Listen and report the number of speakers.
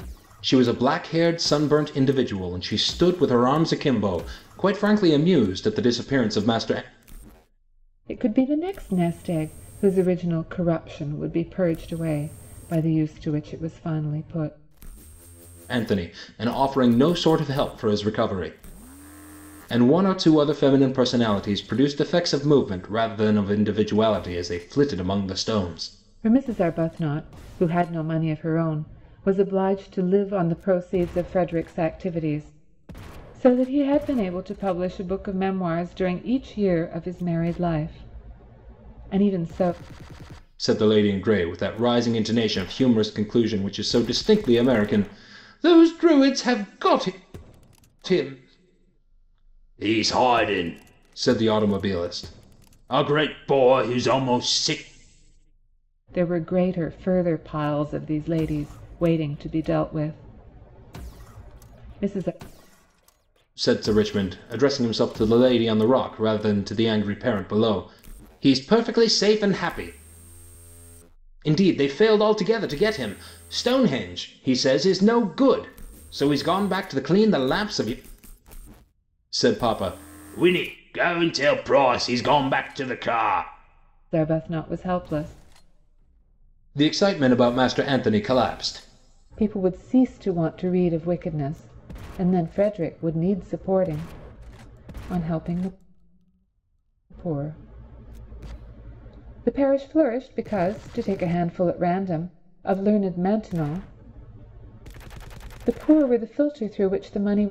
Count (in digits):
2